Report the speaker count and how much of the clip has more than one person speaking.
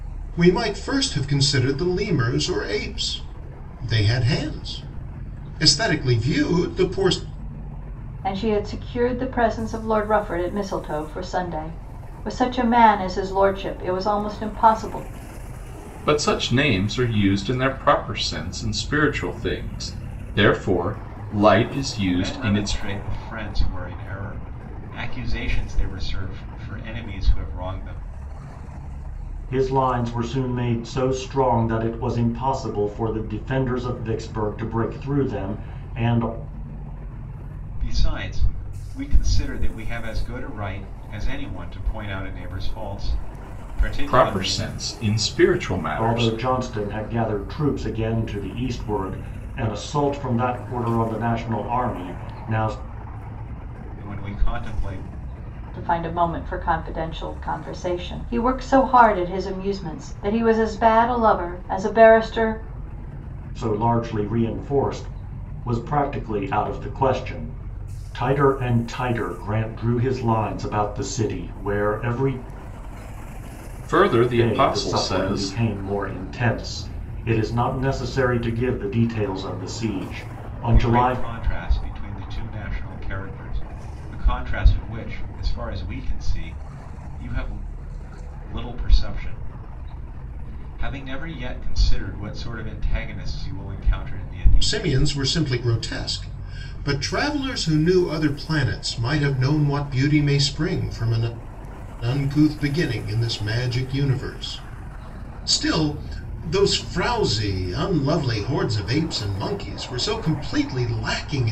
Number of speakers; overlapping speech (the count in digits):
5, about 4%